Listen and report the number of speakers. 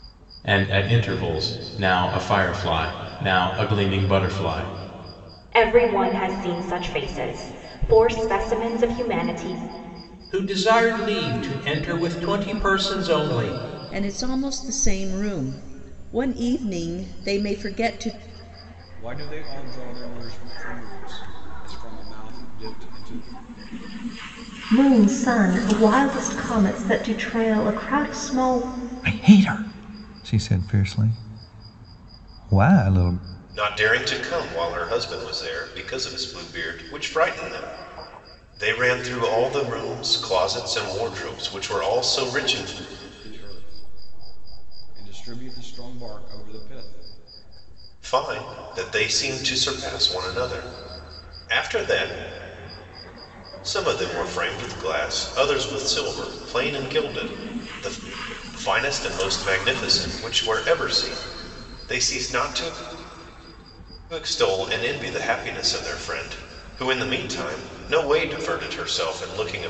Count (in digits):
8